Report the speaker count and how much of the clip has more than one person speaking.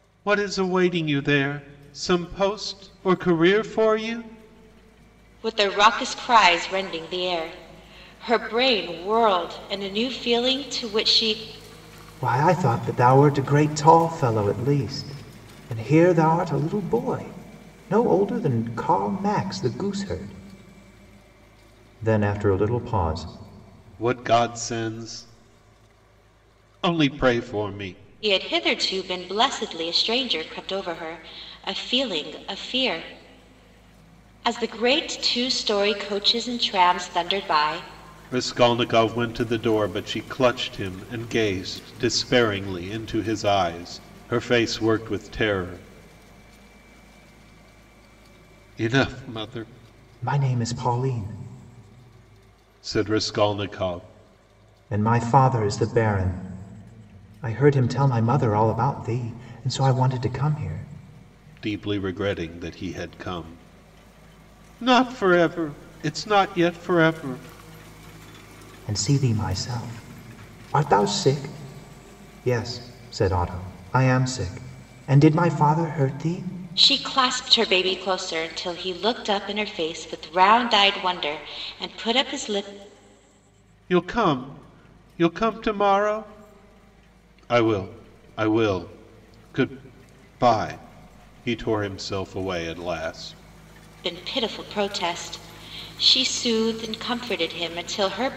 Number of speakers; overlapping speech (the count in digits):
3, no overlap